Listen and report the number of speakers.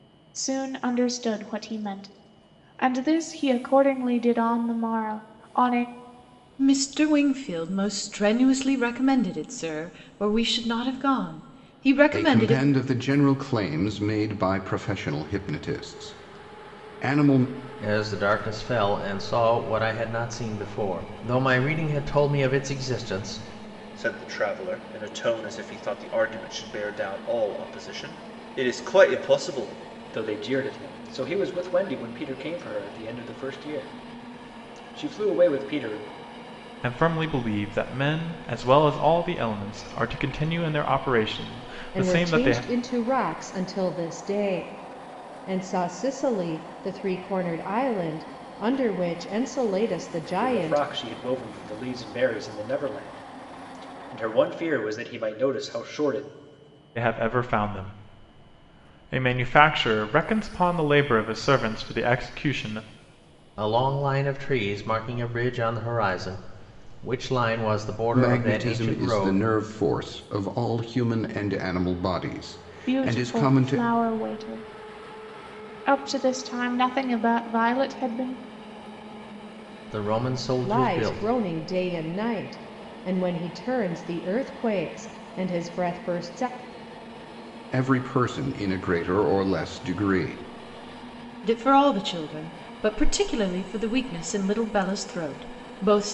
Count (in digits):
8